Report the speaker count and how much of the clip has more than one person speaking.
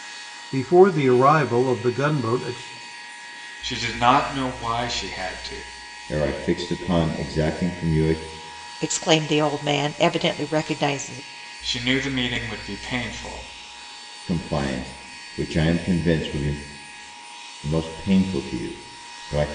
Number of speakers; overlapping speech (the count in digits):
4, no overlap